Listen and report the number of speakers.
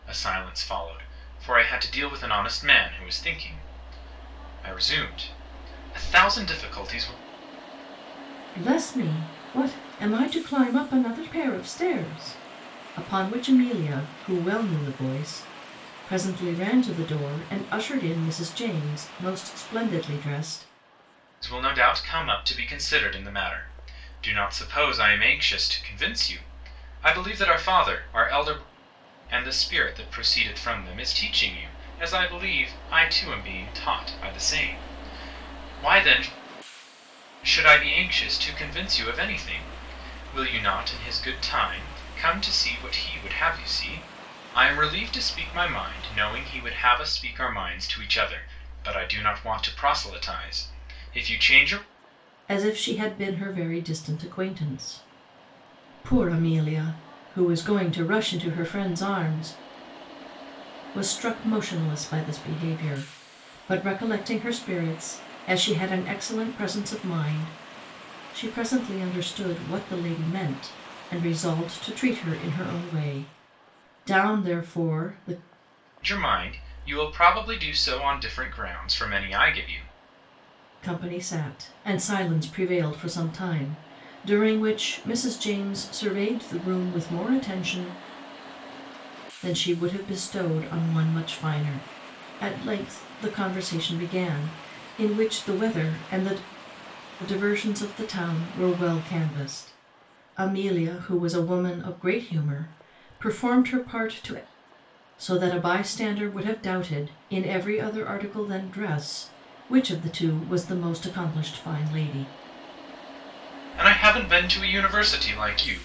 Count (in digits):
2